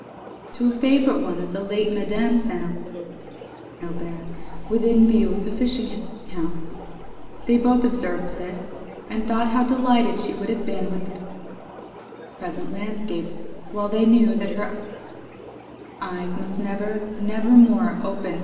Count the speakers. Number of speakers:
1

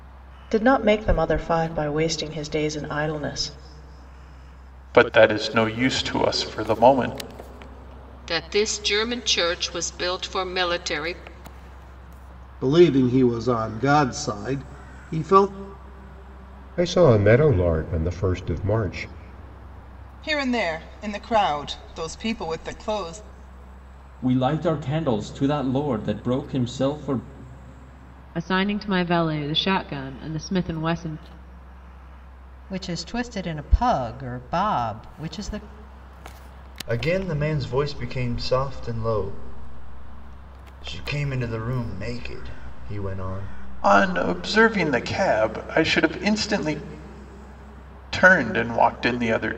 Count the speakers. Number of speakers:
10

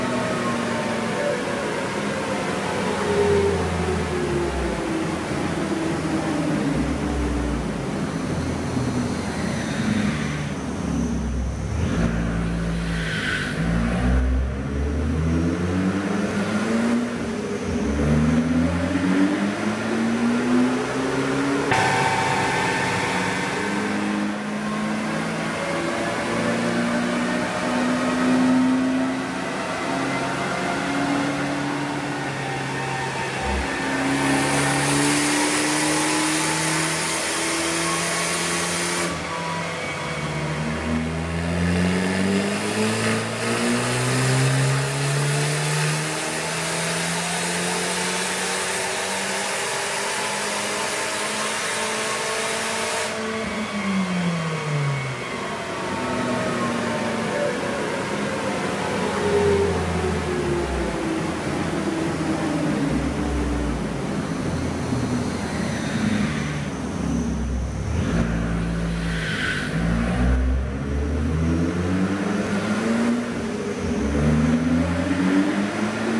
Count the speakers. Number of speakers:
0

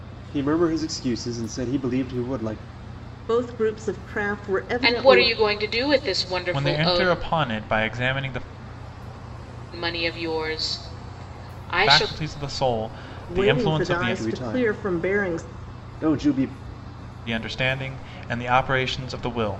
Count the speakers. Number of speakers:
4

